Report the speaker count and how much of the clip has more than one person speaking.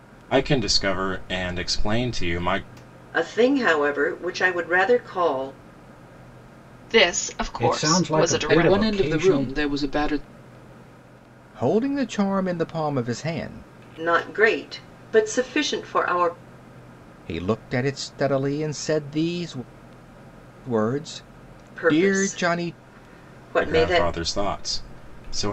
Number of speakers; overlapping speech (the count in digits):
6, about 14%